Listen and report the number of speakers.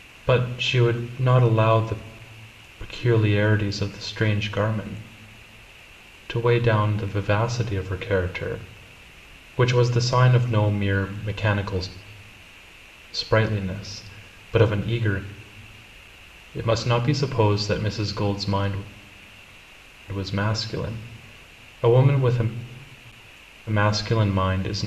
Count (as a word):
one